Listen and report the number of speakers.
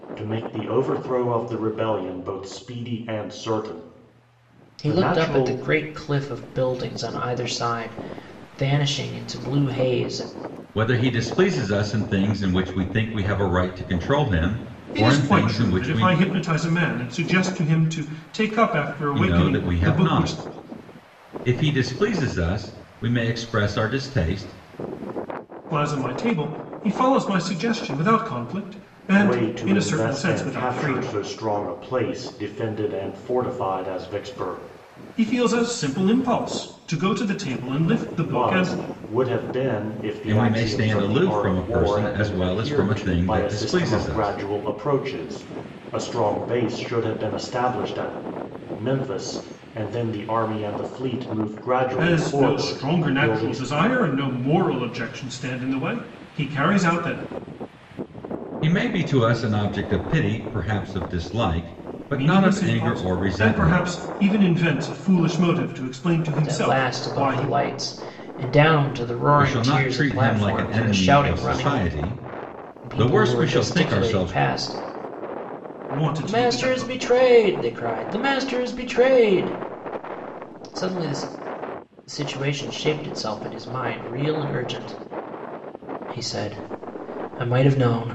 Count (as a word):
four